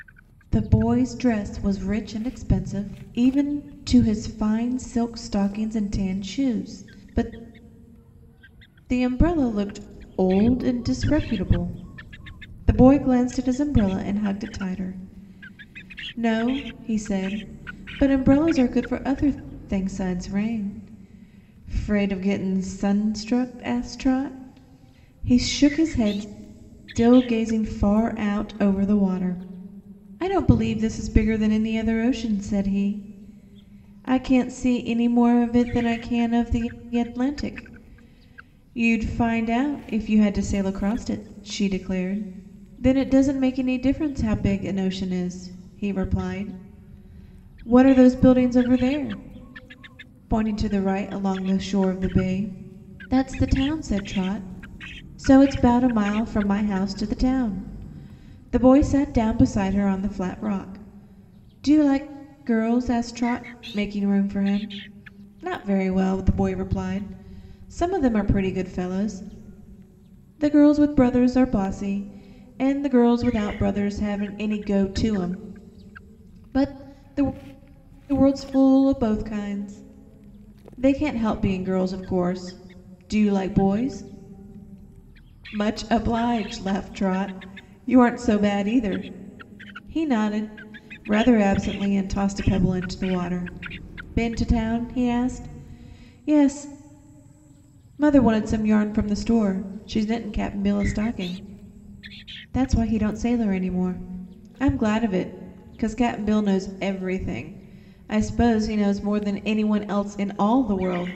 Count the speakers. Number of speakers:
one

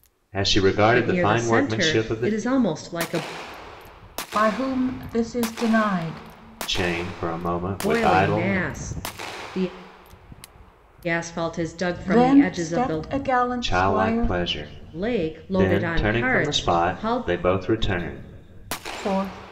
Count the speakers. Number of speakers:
three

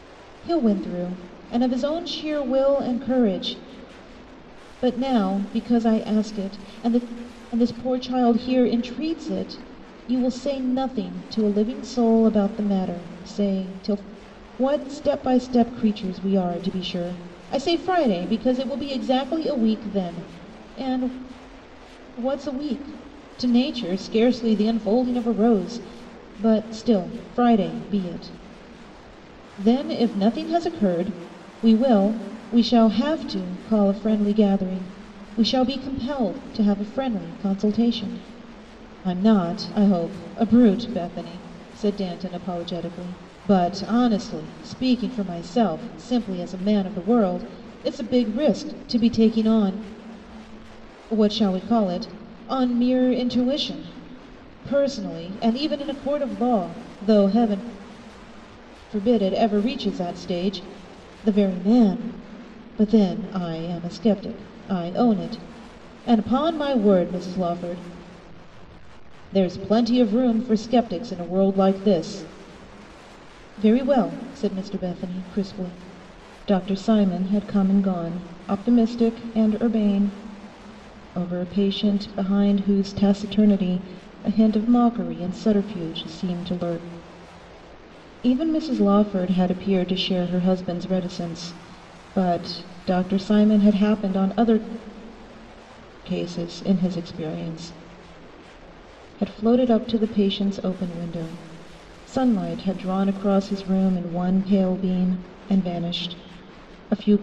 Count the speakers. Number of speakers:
one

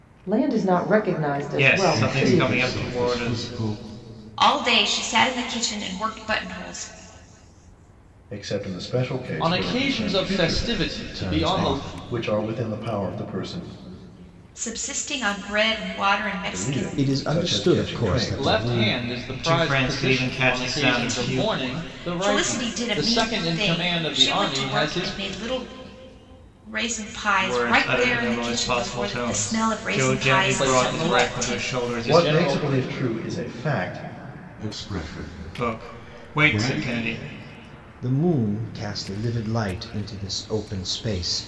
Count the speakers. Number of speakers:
seven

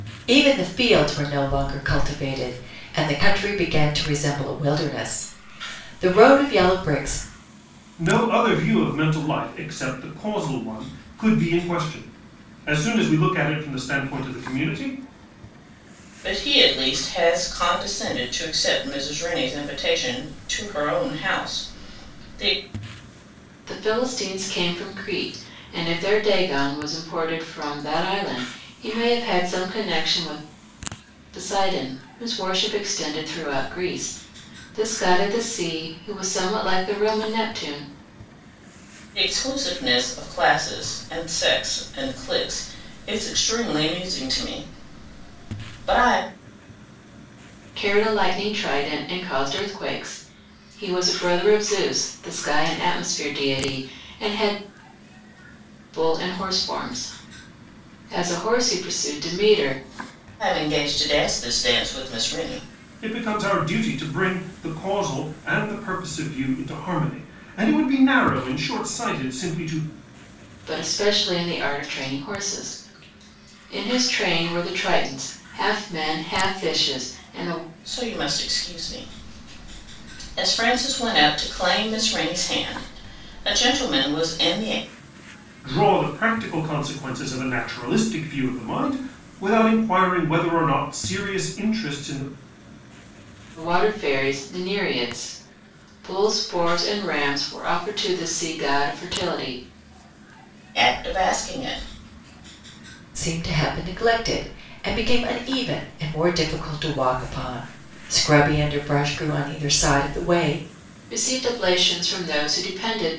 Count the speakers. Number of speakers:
four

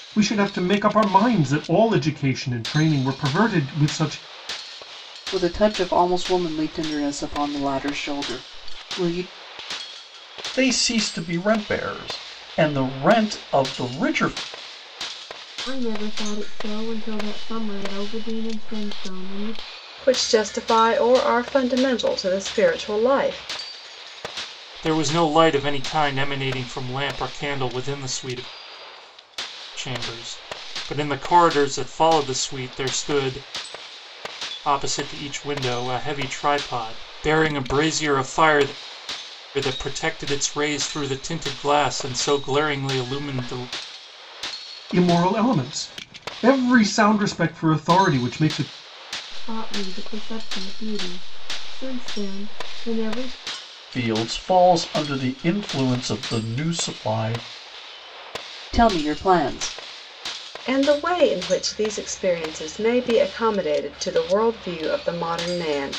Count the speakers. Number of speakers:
six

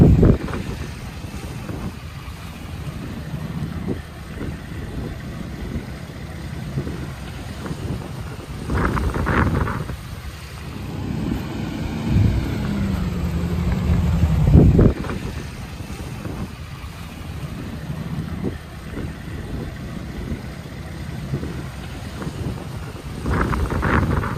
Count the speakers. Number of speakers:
zero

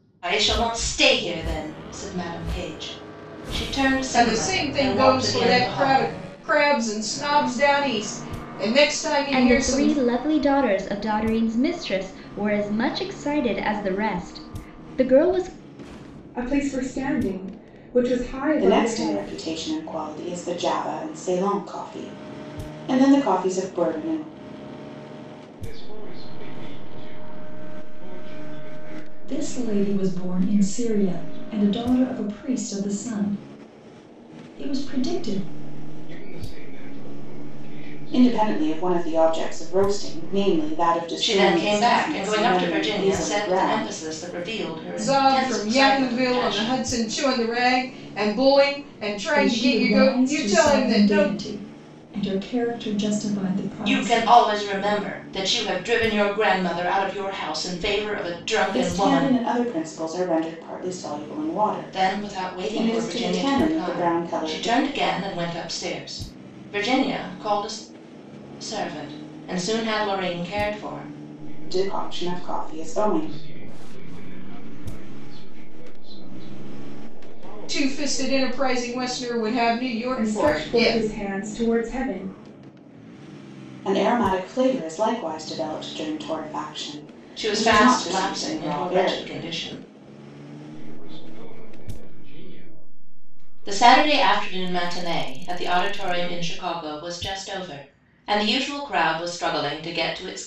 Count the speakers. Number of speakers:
seven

